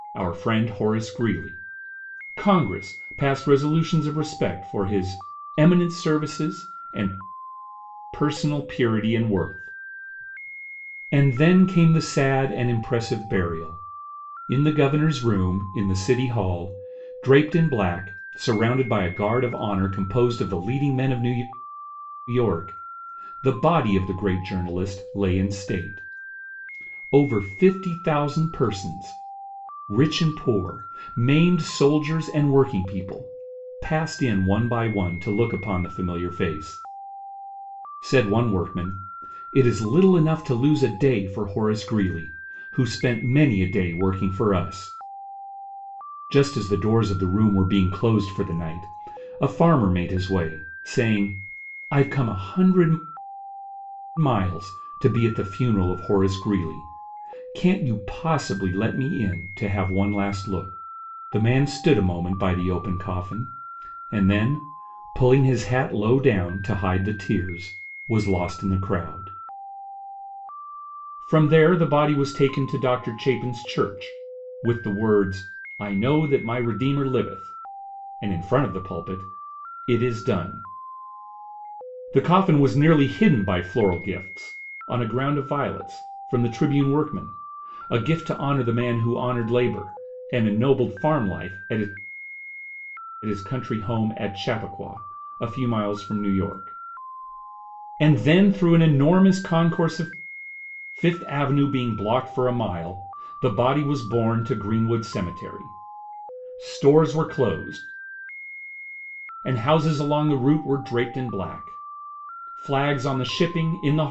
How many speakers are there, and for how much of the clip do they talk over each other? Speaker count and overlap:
one, no overlap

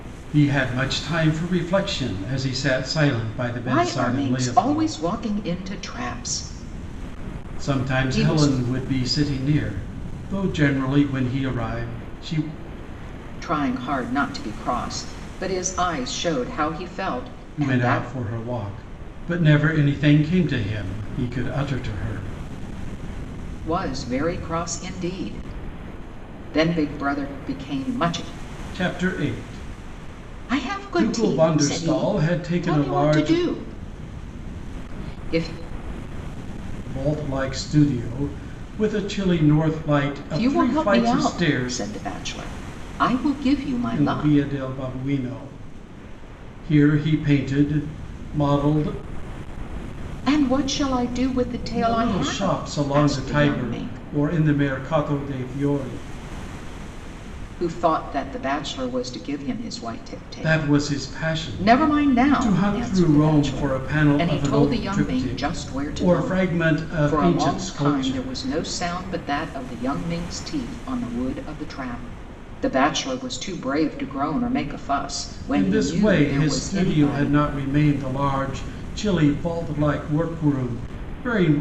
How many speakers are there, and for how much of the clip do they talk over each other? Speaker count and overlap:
two, about 25%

